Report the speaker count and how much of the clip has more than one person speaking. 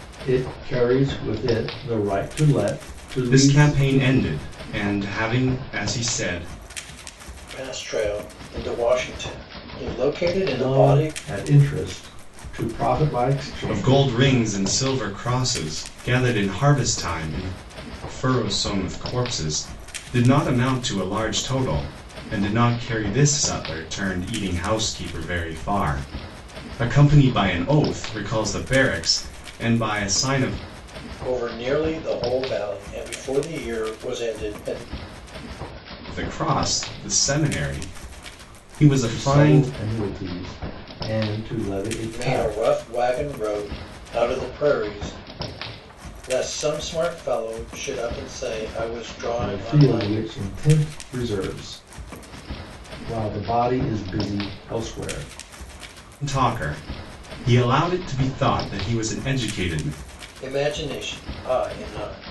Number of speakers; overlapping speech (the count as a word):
three, about 6%